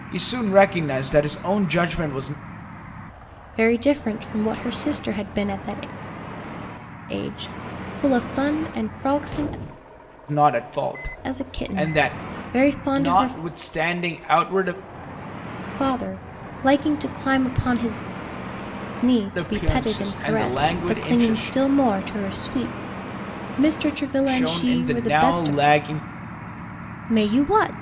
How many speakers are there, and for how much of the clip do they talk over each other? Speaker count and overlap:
two, about 18%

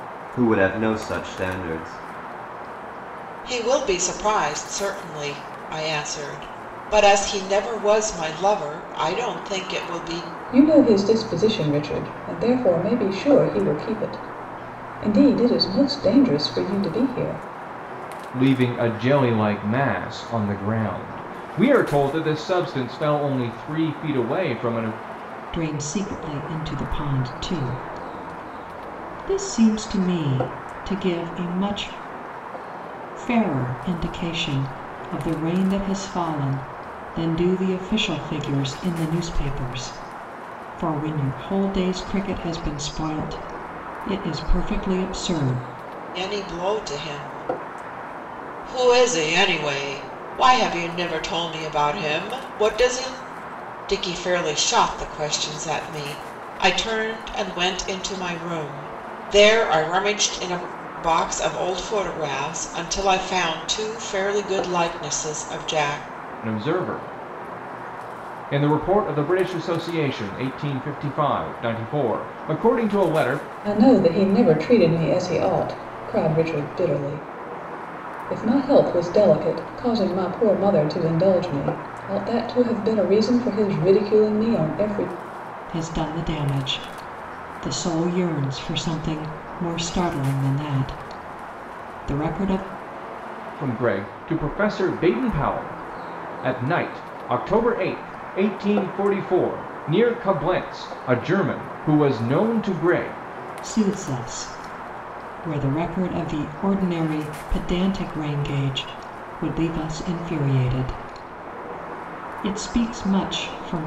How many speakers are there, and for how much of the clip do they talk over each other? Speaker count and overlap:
five, no overlap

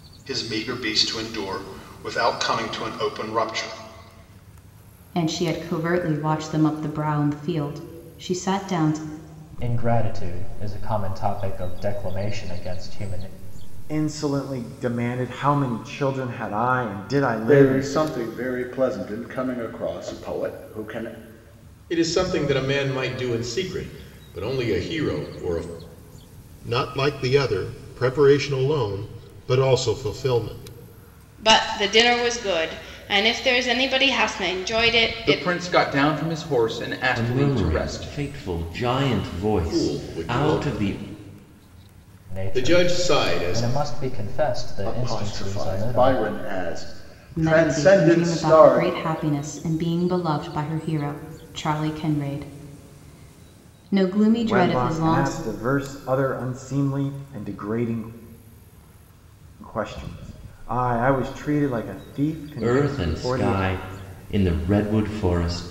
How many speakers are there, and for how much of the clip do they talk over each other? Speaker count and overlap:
ten, about 14%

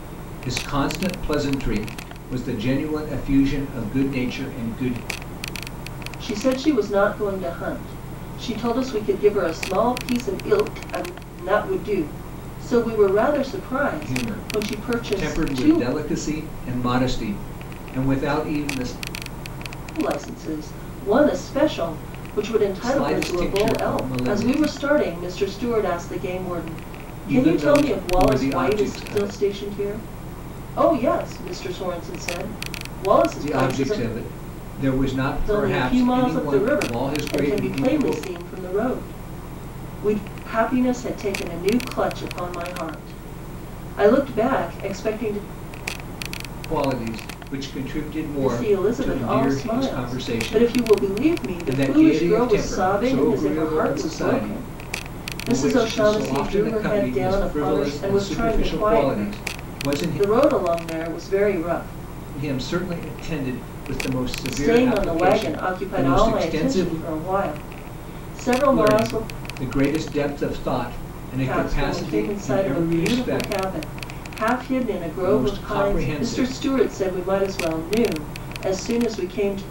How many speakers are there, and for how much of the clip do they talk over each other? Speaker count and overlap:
two, about 33%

